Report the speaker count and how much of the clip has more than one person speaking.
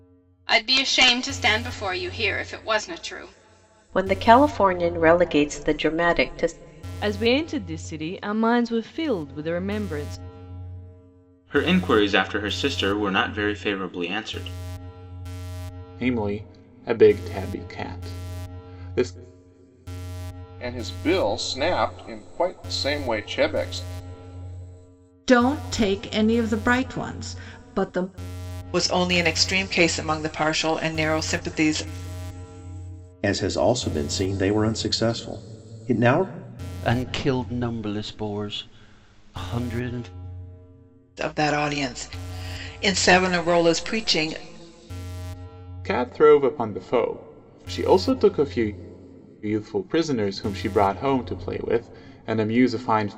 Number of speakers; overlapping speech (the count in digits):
10, no overlap